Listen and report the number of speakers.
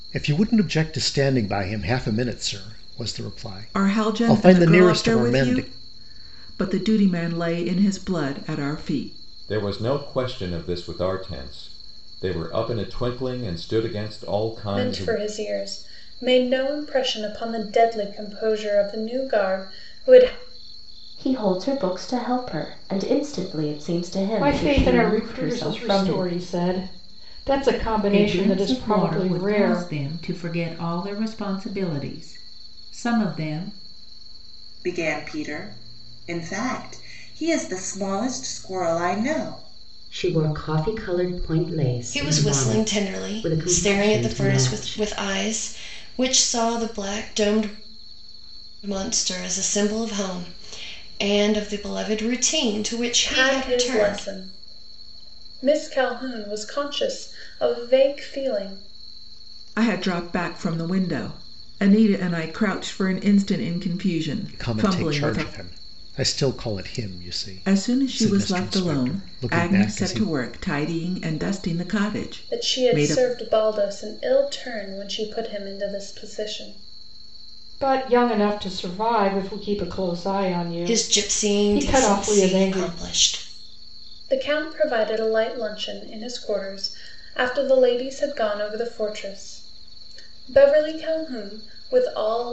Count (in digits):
10